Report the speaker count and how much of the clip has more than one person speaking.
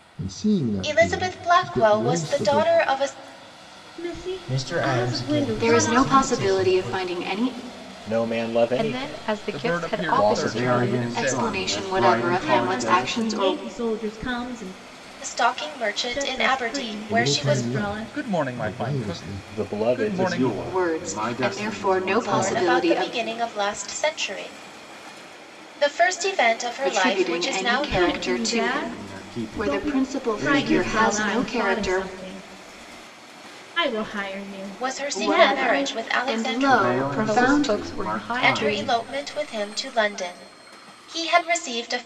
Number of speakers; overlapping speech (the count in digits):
9, about 62%